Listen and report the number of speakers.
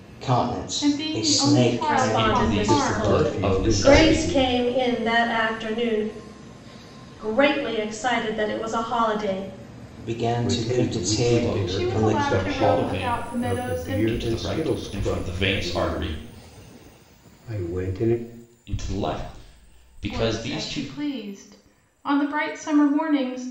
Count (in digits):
5